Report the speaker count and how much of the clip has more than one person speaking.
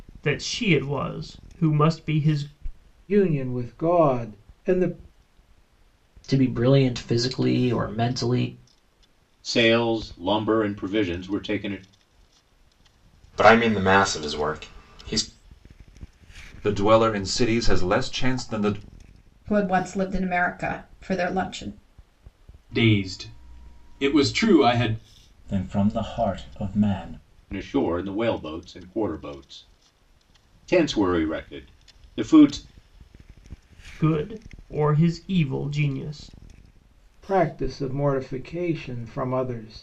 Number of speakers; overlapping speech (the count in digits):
9, no overlap